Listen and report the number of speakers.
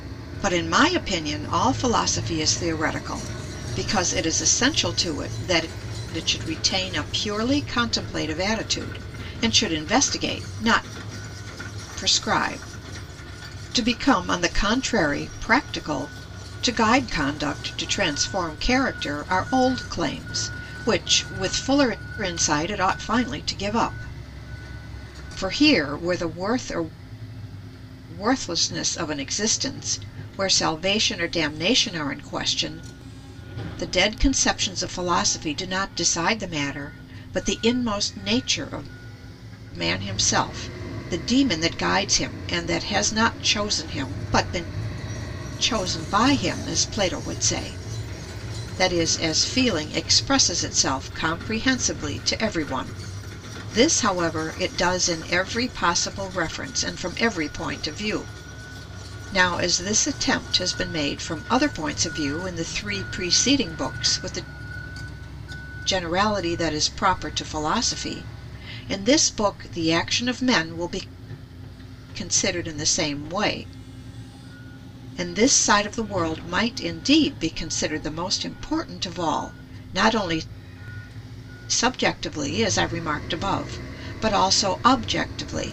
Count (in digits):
1